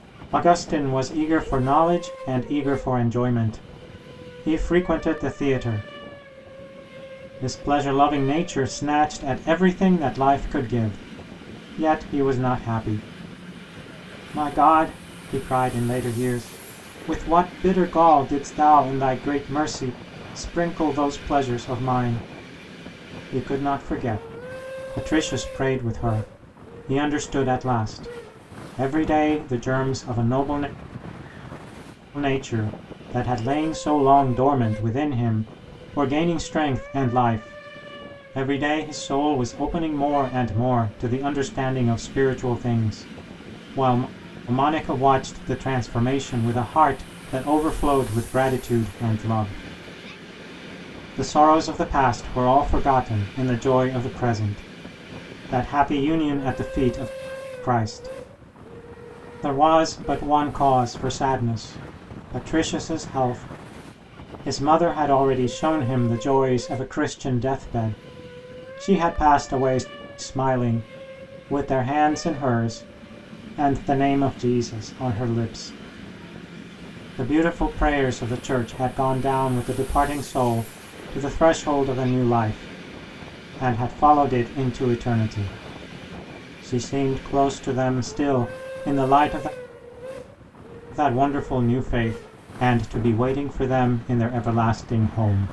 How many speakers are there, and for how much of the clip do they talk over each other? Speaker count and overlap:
one, no overlap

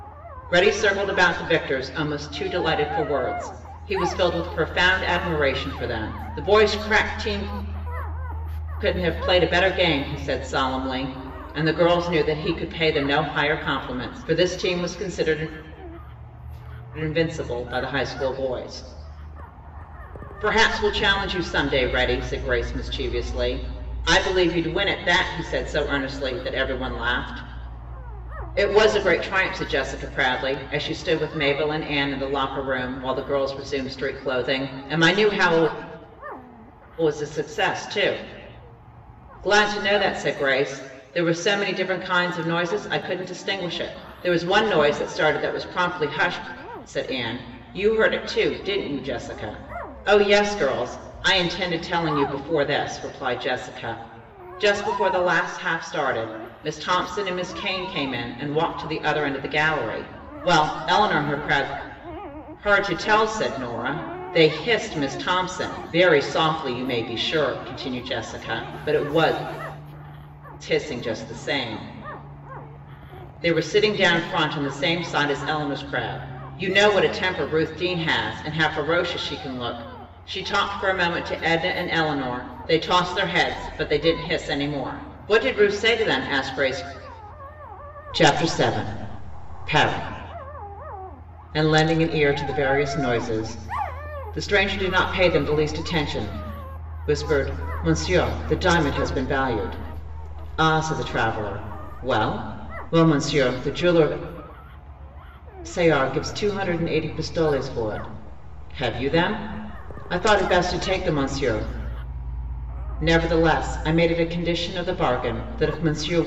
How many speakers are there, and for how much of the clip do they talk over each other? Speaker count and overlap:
one, no overlap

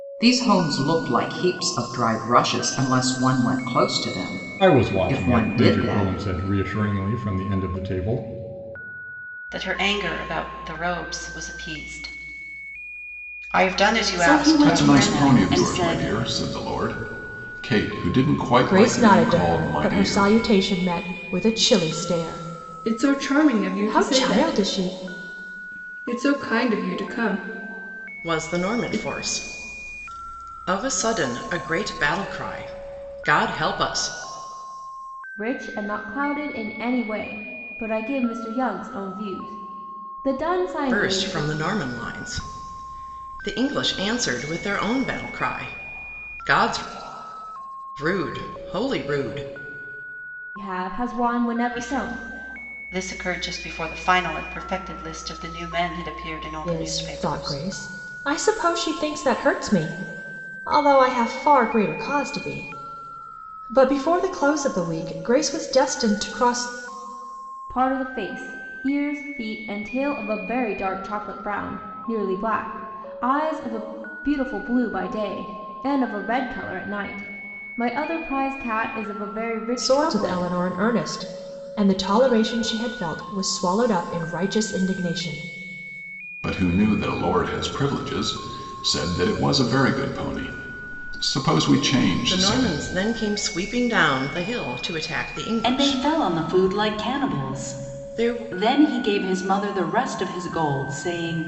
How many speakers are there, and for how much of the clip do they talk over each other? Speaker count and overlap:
nine, about 14%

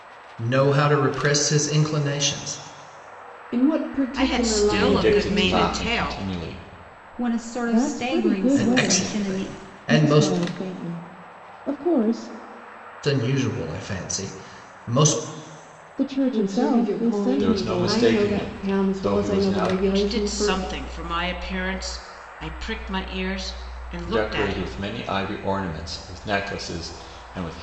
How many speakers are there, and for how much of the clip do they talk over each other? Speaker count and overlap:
six, about 36%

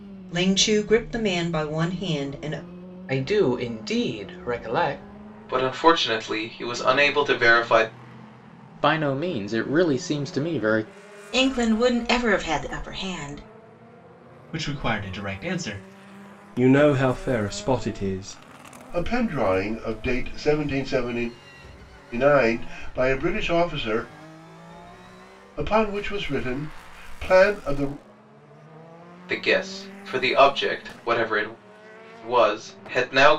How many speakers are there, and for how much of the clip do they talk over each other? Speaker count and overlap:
eight, no overlap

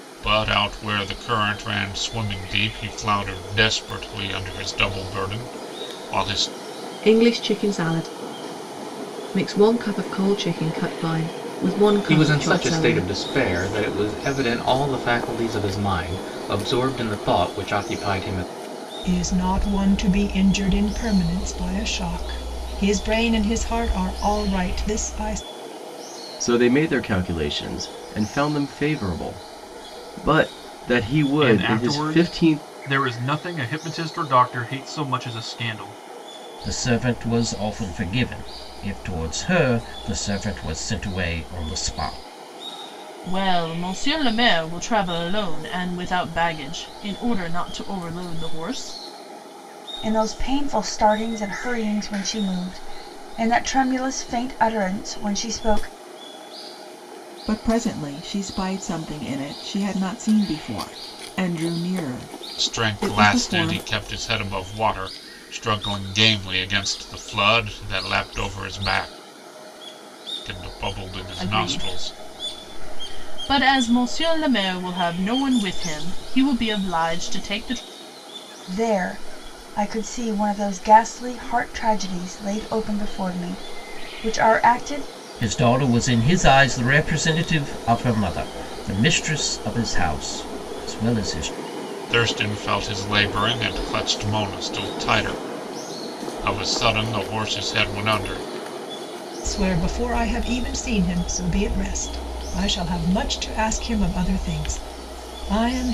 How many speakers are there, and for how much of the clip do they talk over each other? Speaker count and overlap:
ten, about 4%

